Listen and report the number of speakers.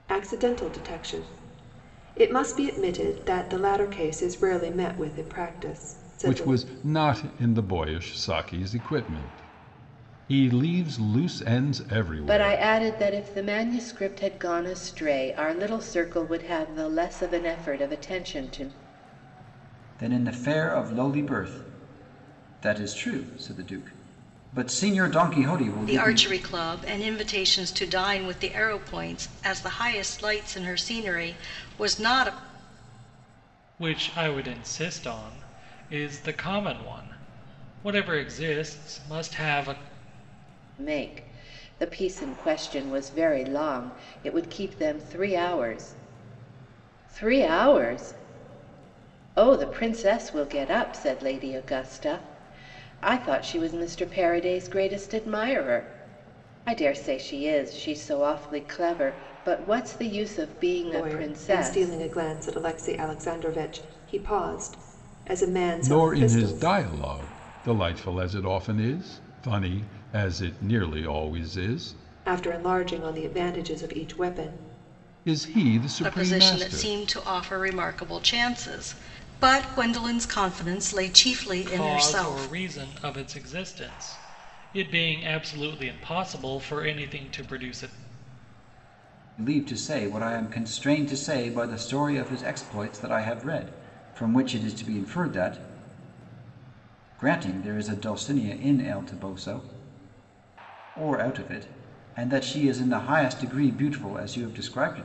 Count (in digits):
6